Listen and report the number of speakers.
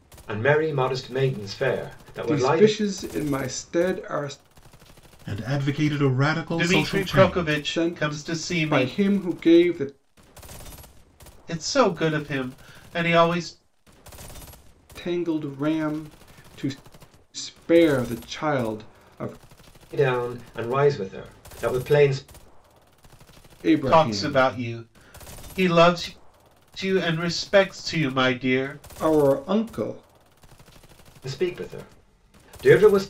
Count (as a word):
four